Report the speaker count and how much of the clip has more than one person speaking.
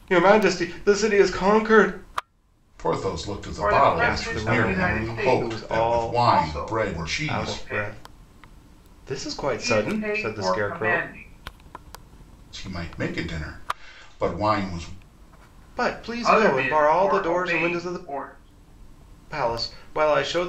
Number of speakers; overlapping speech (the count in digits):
3, about 38%